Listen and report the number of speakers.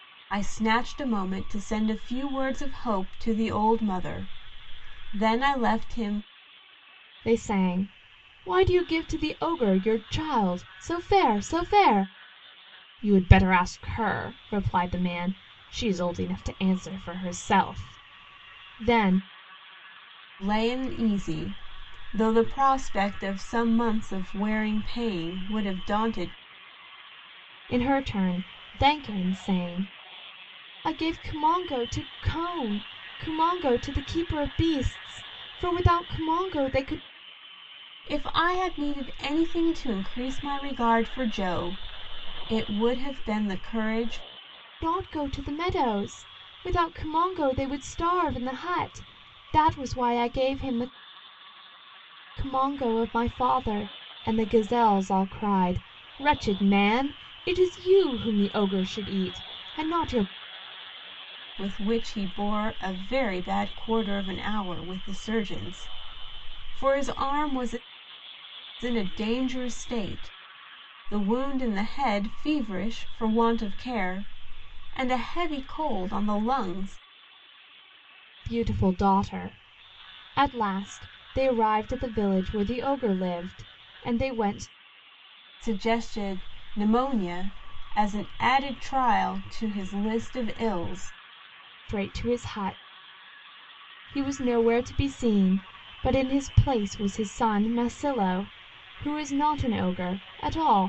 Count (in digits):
2